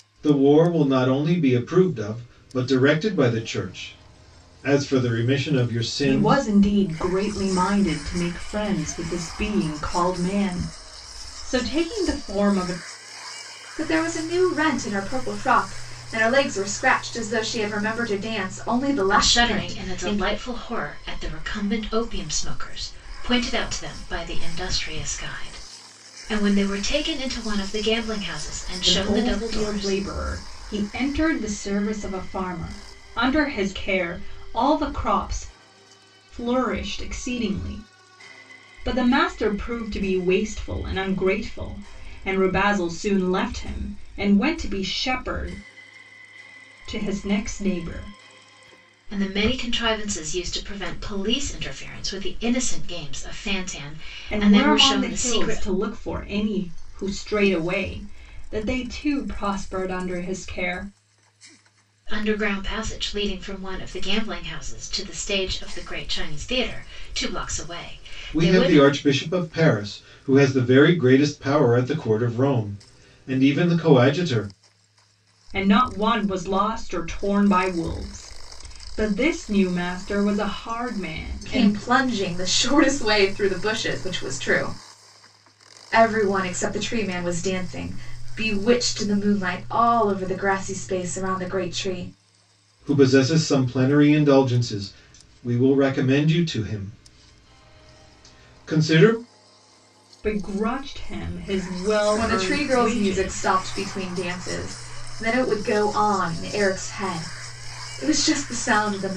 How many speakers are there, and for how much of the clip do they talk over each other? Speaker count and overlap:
4, about 6%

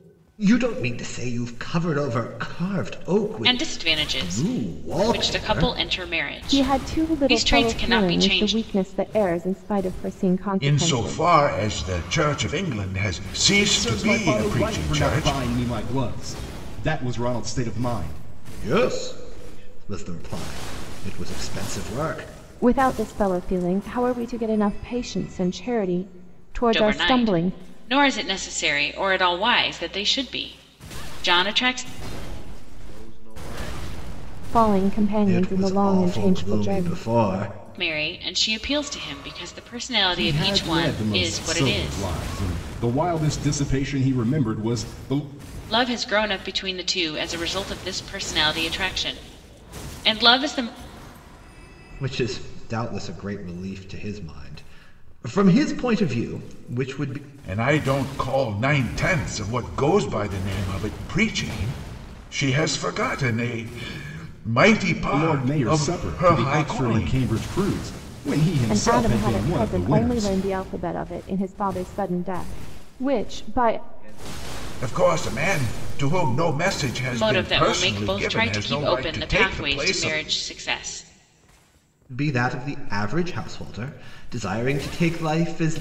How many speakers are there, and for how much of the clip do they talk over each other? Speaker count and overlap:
6, about 33%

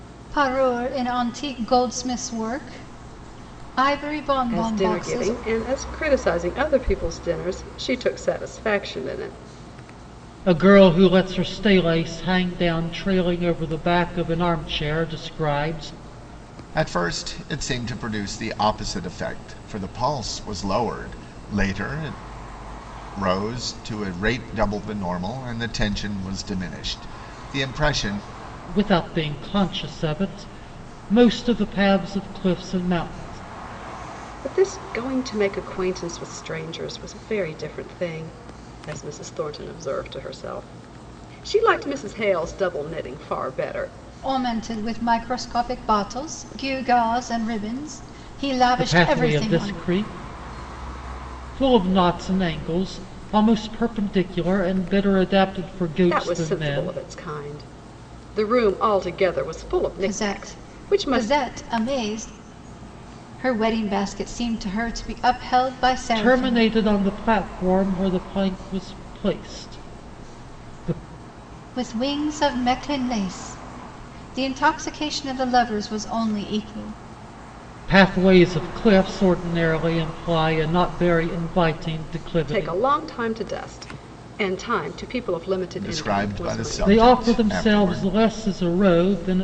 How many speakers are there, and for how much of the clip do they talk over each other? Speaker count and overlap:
4, about 8%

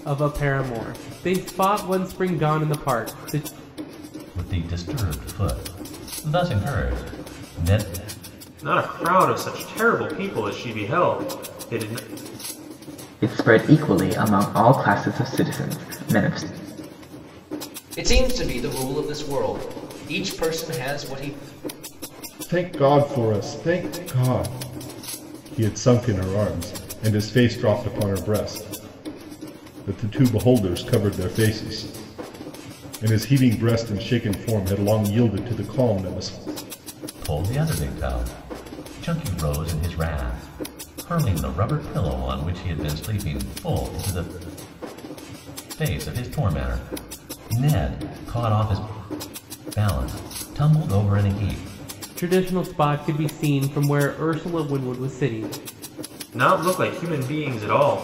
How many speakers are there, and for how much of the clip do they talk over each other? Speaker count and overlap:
6, no overlap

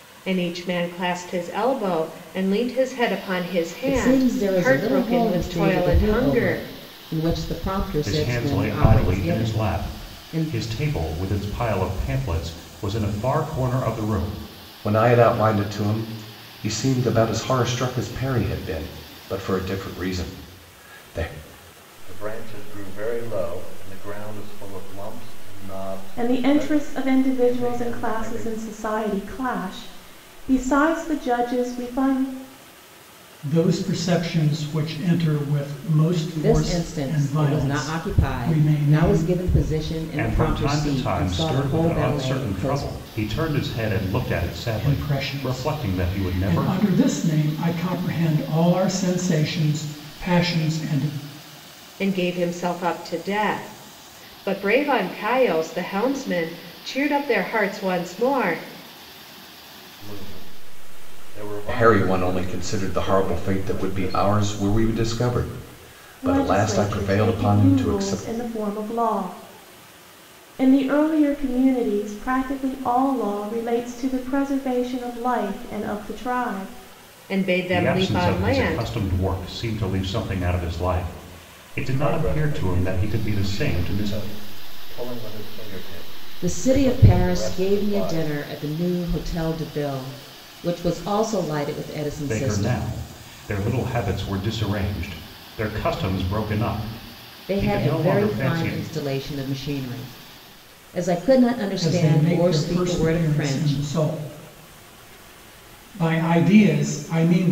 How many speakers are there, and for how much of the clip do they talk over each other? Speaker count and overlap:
7, about 28%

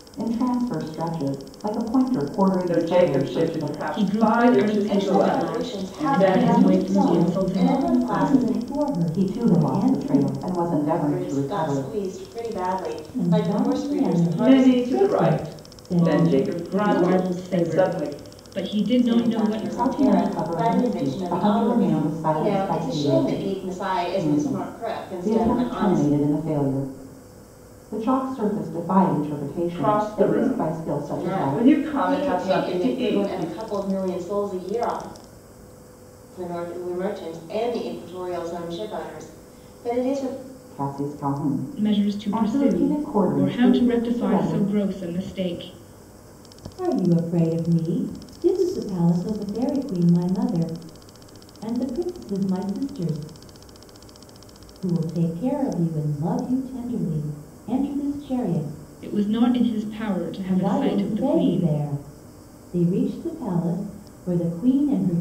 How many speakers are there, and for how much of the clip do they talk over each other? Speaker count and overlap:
5, about 43%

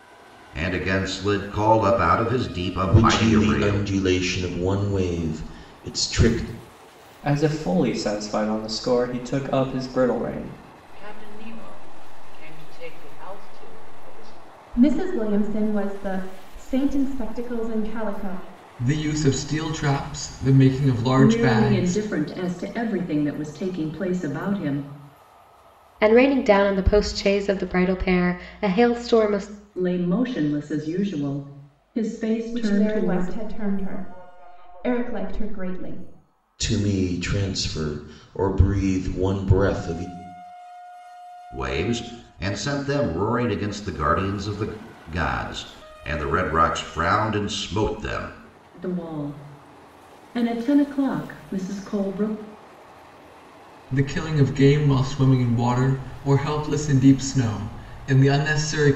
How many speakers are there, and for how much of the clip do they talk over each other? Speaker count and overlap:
8, about 5%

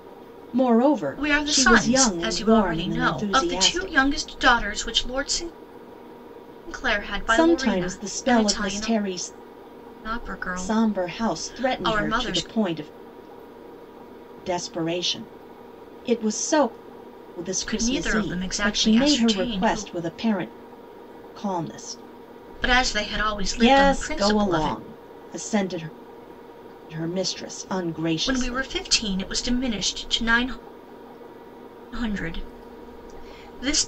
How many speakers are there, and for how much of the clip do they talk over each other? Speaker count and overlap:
2, about 31%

